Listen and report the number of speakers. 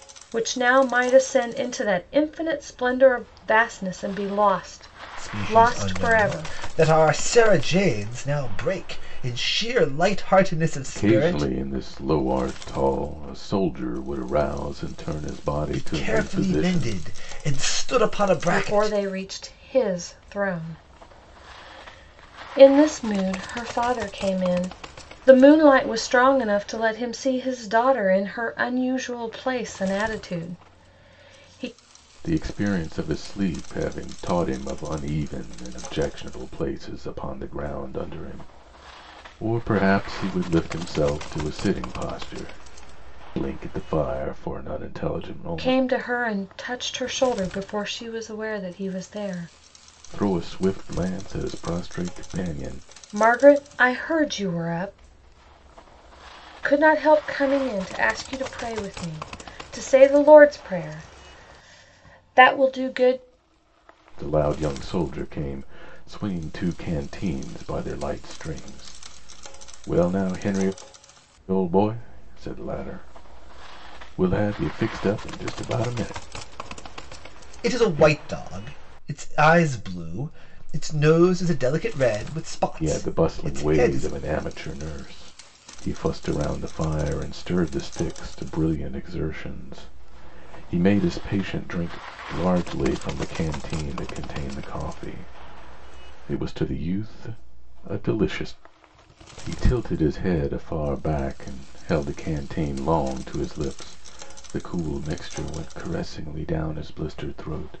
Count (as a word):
three